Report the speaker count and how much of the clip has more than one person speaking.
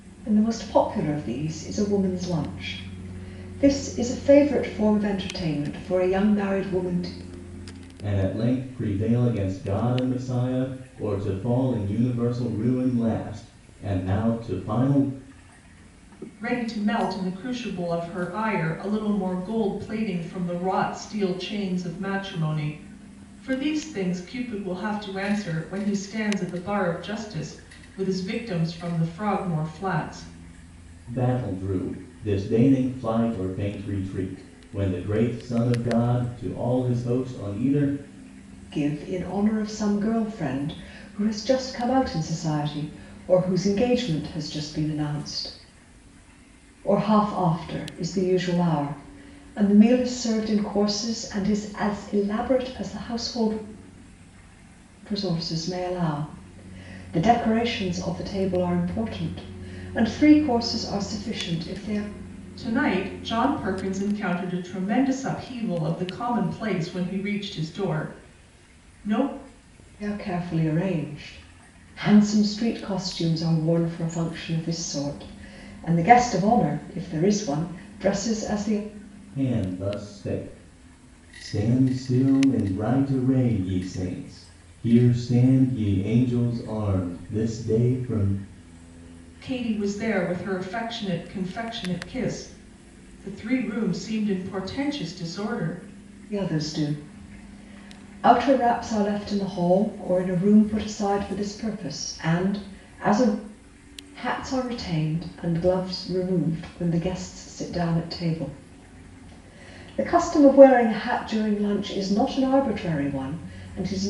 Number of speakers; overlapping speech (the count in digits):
3, no overlap